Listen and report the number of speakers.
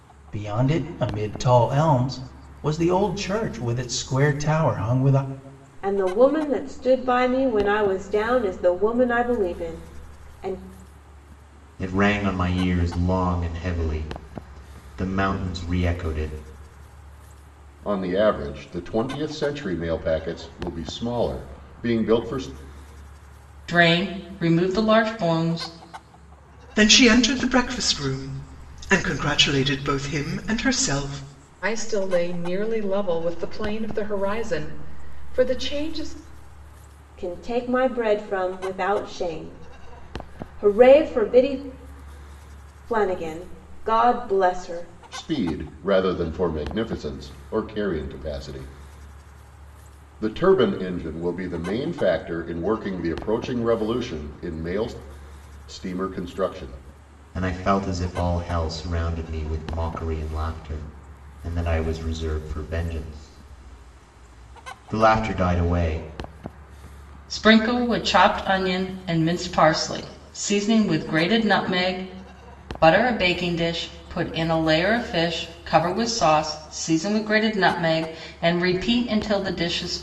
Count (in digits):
7